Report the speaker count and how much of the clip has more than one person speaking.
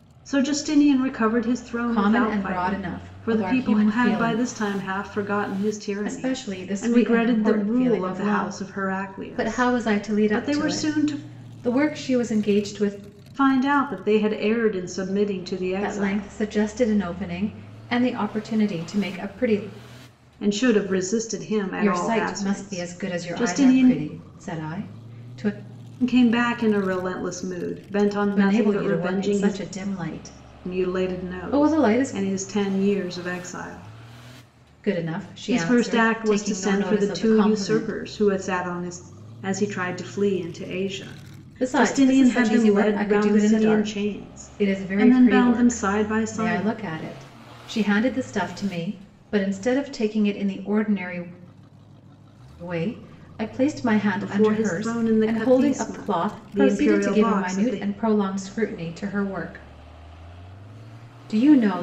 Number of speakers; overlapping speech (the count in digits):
2, about 39%